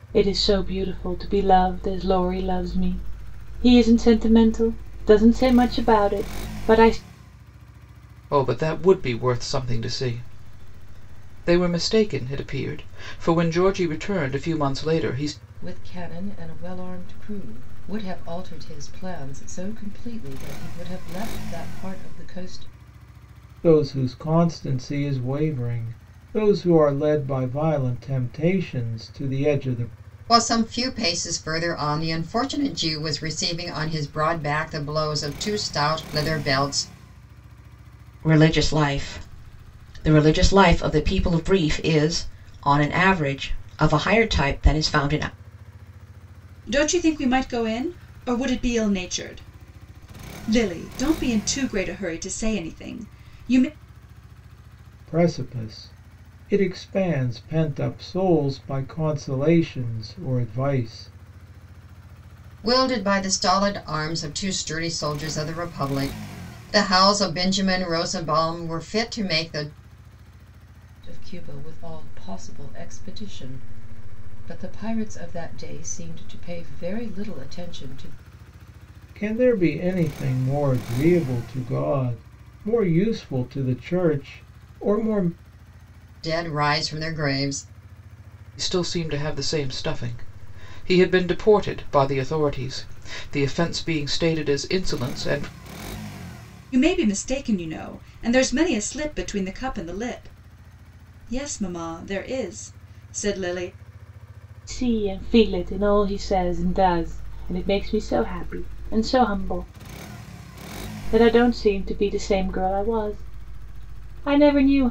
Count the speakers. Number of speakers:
seven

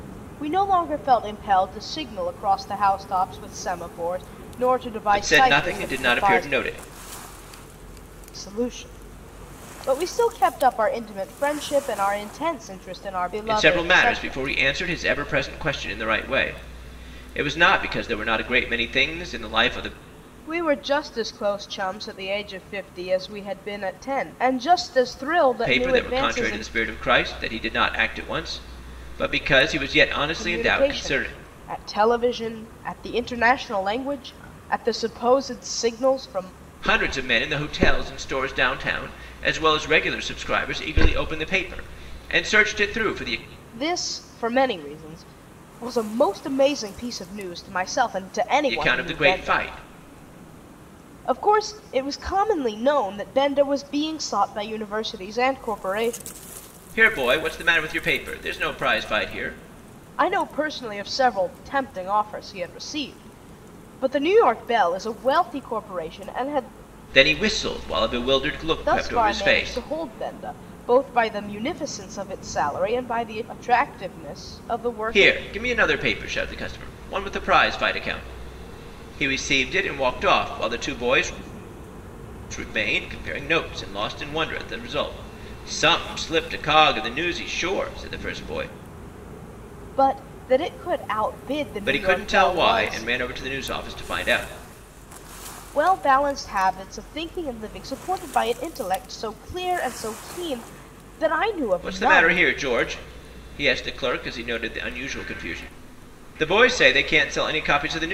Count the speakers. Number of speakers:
two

